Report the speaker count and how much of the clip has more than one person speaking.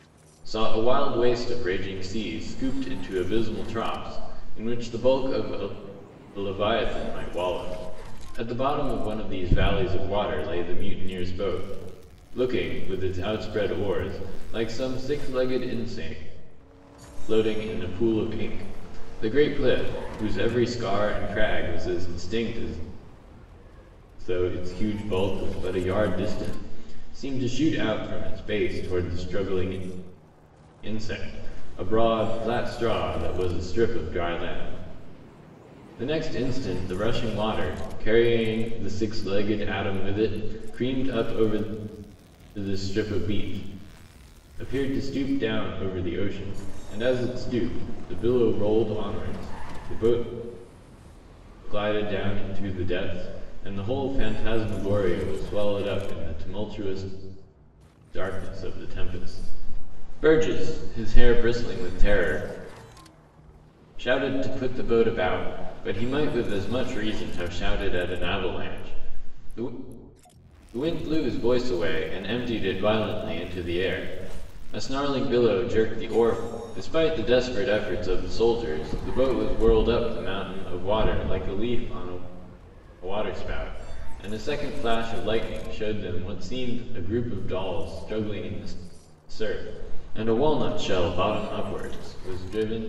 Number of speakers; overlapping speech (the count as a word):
one, no overlap